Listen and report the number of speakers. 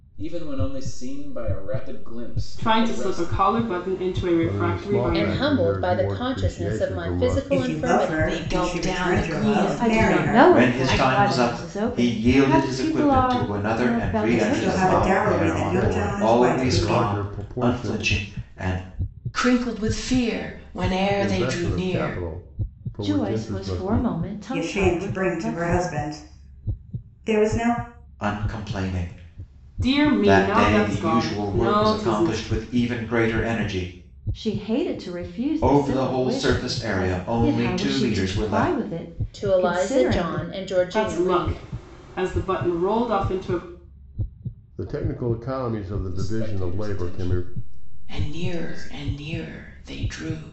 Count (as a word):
eight